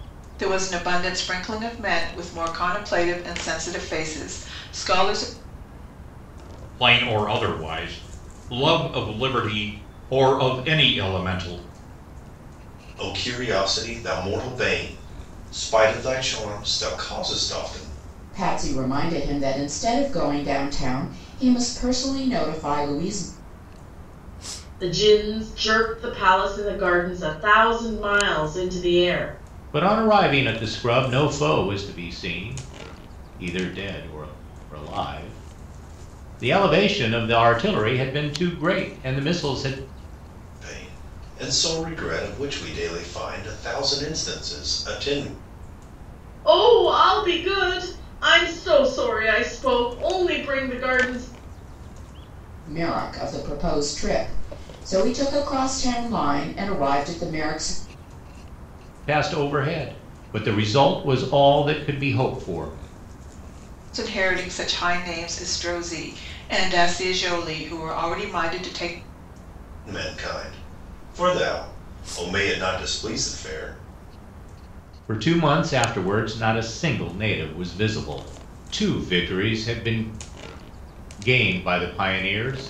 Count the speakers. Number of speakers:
6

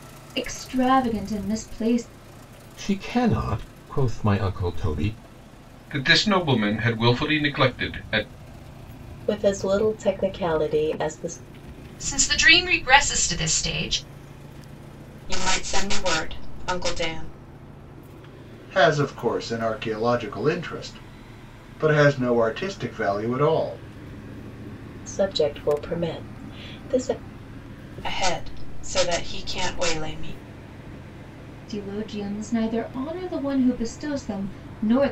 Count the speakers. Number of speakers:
7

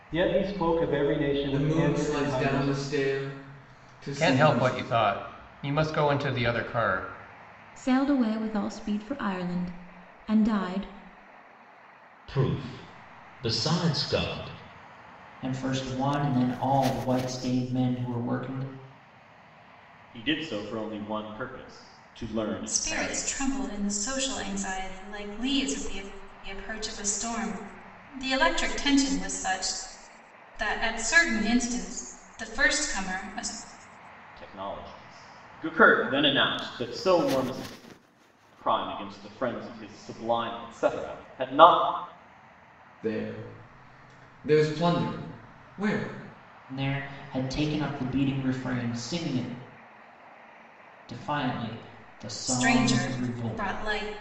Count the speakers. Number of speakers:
8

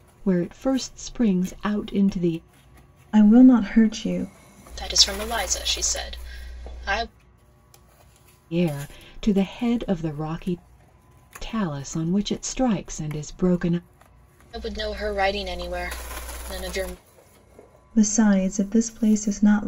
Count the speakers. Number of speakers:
3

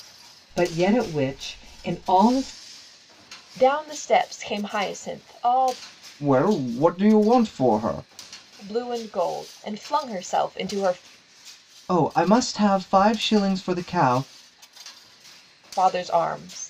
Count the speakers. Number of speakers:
3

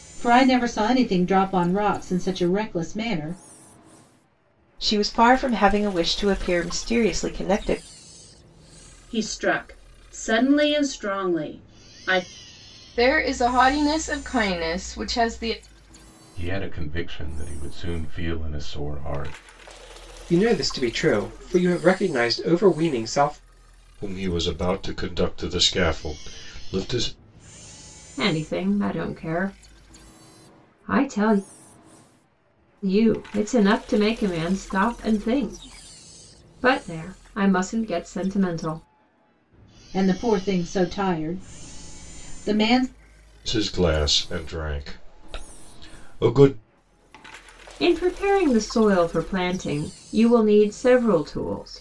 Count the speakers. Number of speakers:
8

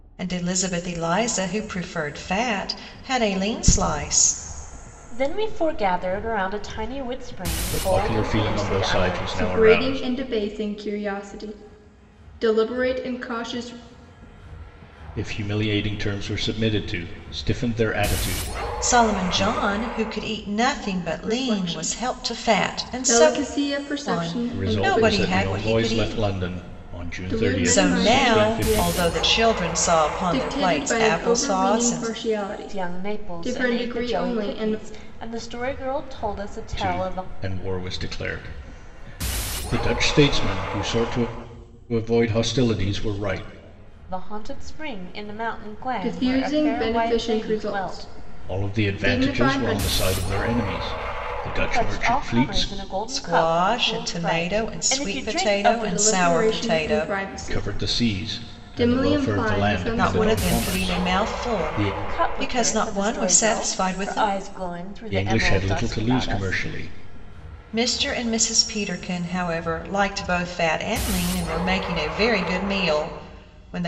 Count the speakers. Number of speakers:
4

